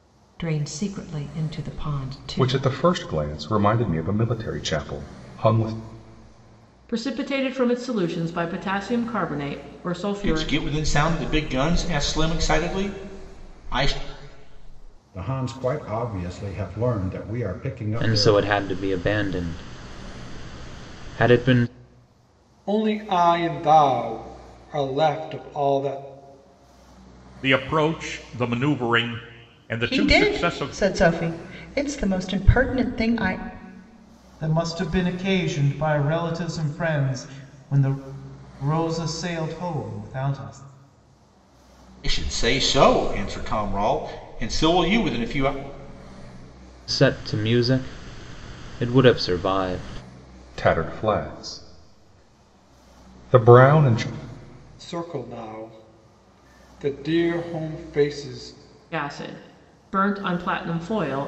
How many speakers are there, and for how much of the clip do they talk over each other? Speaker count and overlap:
ten, about 4%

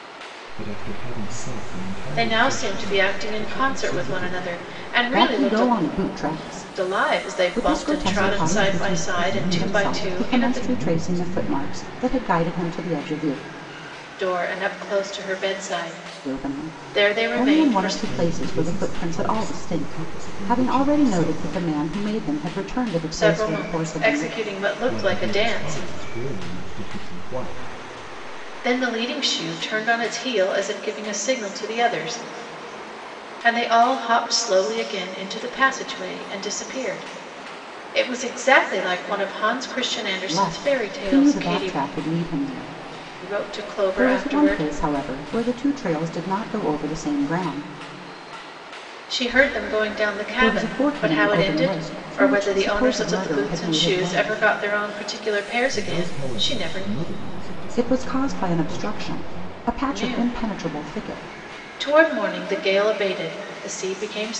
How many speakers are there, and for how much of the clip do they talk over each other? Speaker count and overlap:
three, about 41%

